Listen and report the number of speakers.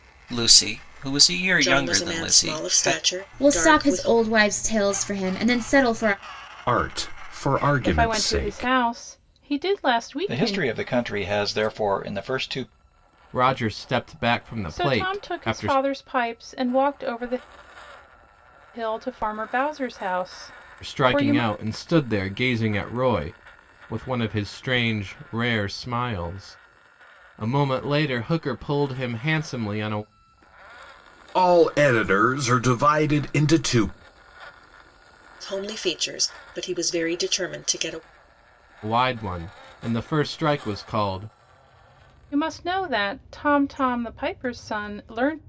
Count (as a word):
seven